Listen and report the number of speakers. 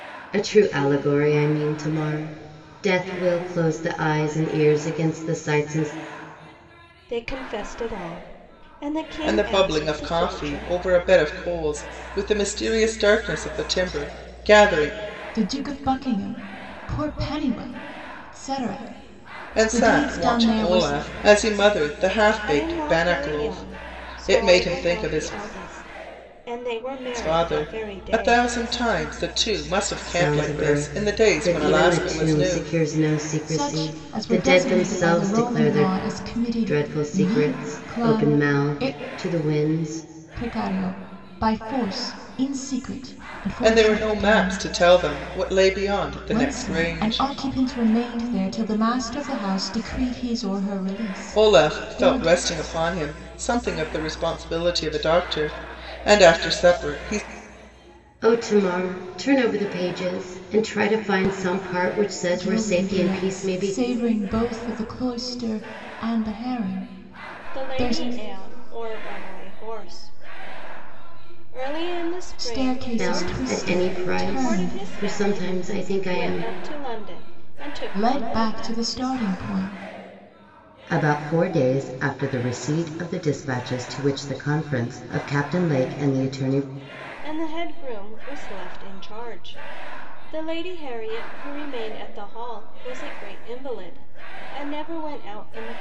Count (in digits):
4